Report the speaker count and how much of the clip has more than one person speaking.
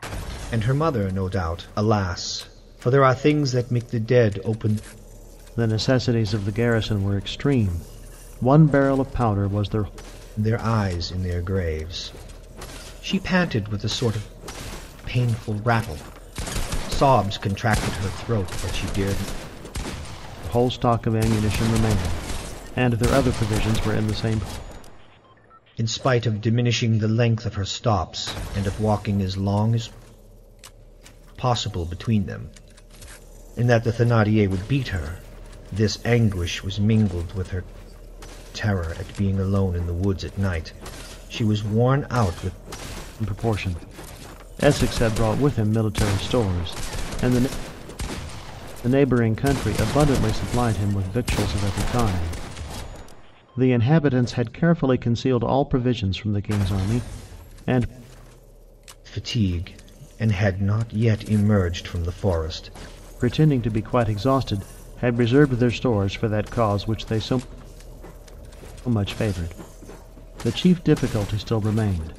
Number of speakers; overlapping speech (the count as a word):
two, no overlap